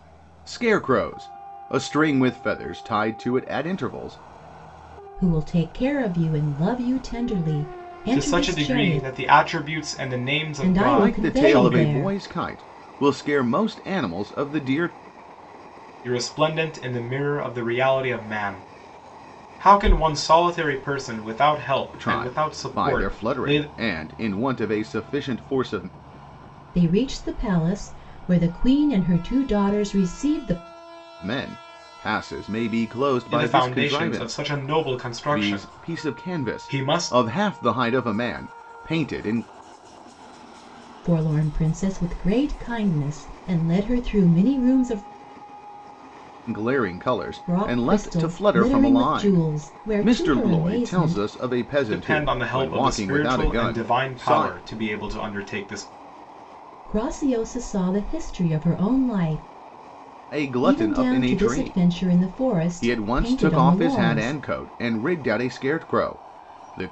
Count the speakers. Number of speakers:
3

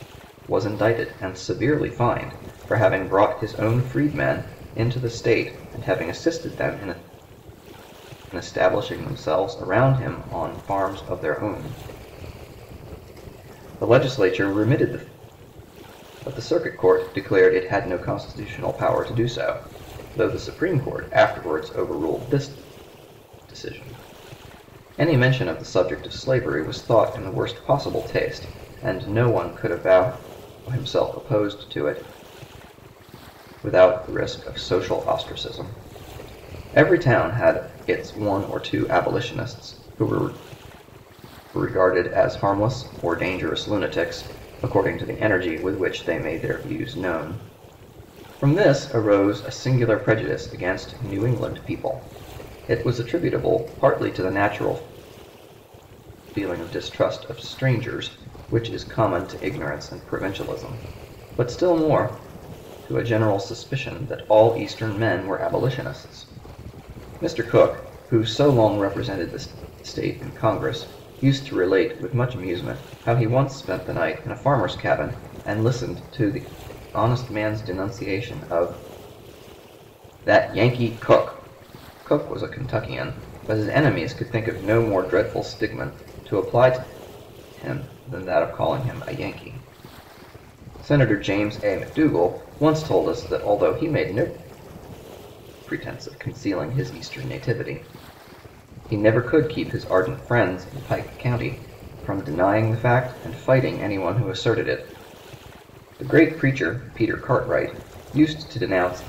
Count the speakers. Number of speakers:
1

